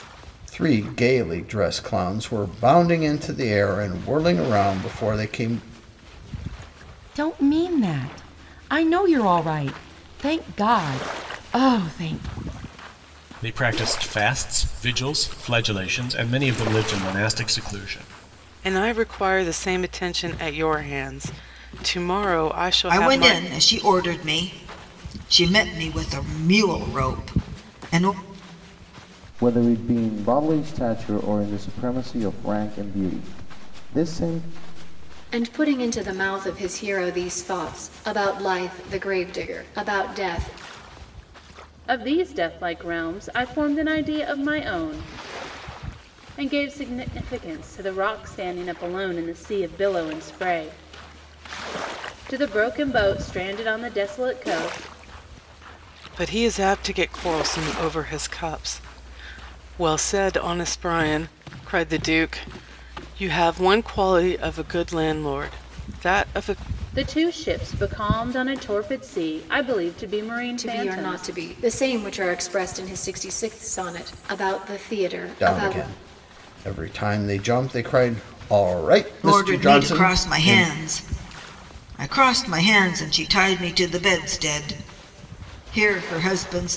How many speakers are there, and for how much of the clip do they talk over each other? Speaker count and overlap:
eight, about 4%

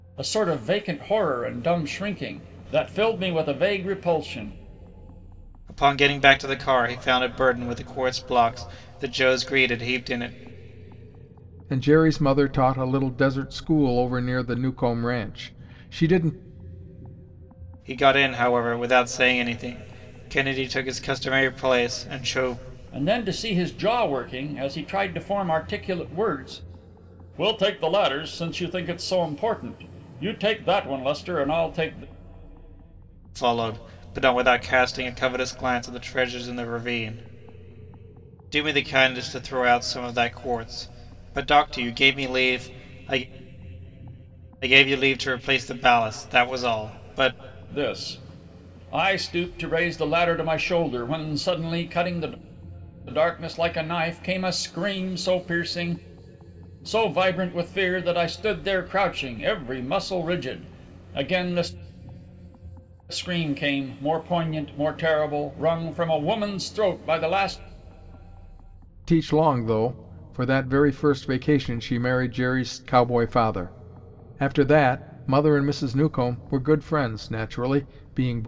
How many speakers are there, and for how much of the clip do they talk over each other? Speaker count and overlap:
three, no overlap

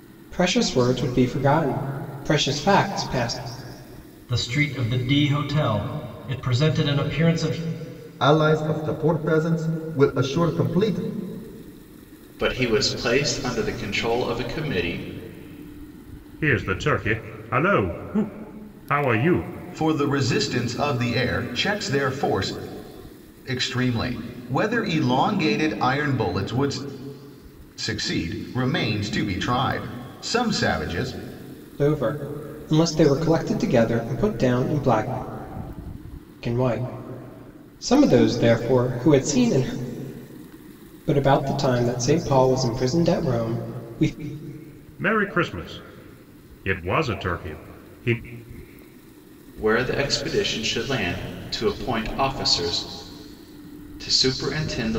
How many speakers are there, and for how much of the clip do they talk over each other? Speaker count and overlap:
six, no overlap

